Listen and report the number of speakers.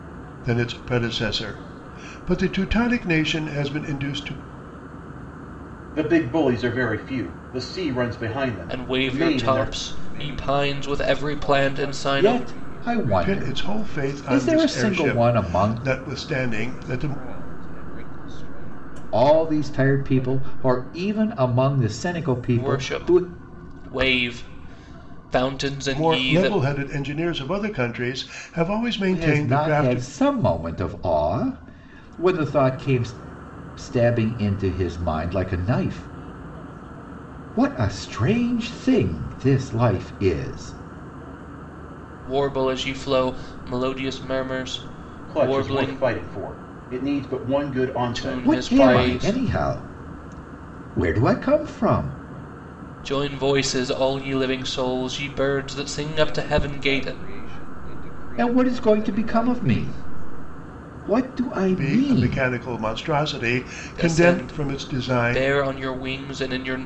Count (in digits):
5